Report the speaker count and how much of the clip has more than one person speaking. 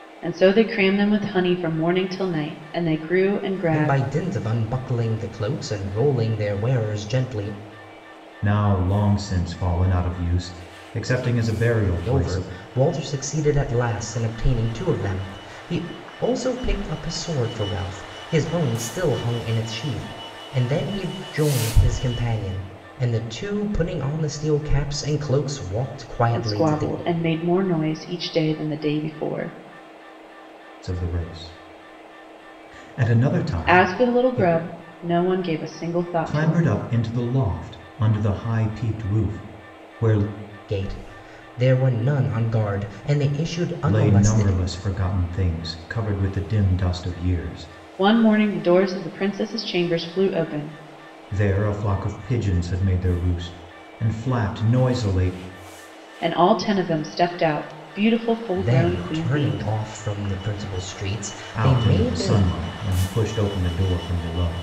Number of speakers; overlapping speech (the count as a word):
three, about 9%